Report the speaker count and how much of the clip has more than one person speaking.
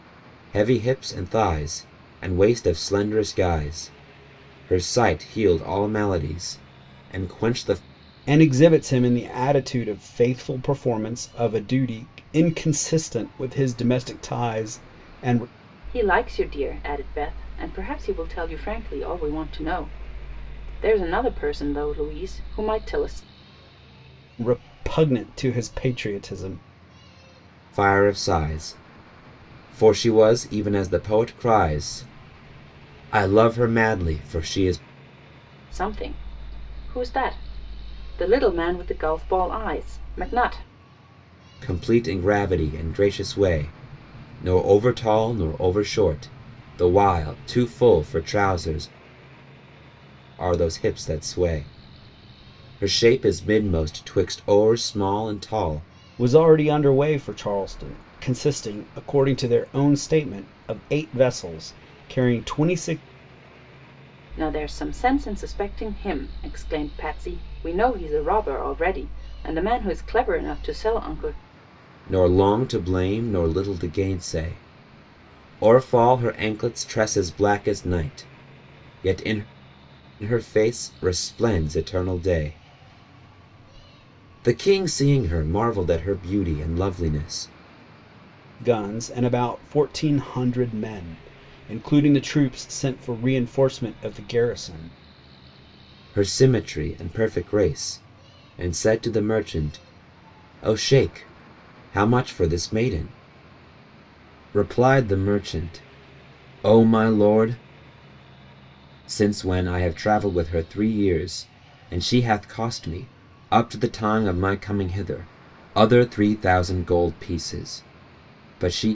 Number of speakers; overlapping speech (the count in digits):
3, no overlap